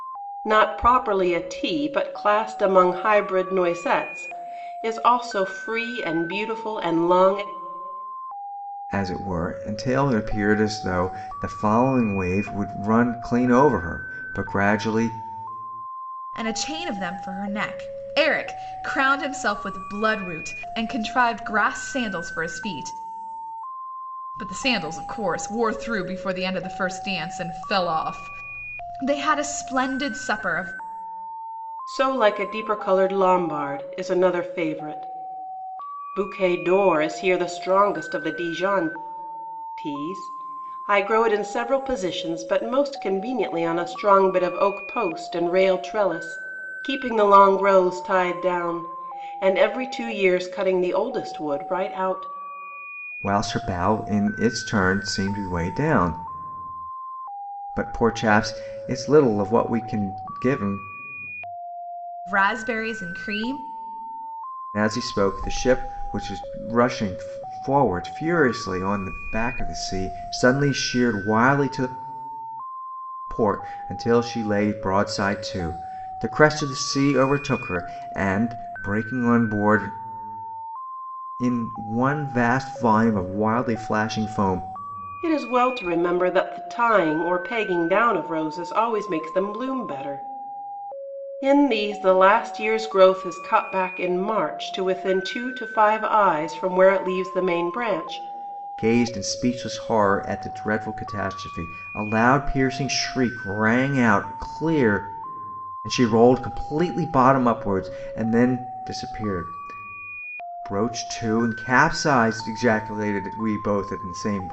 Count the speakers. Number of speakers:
3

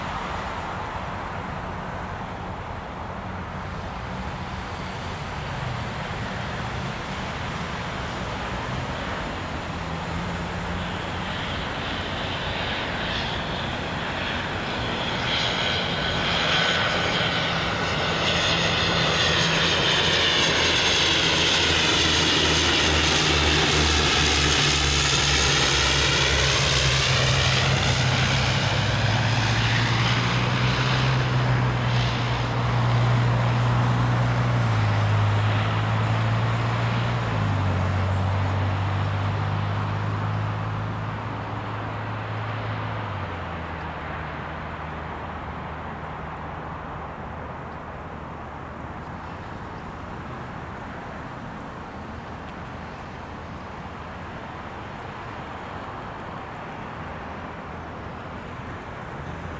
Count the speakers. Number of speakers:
0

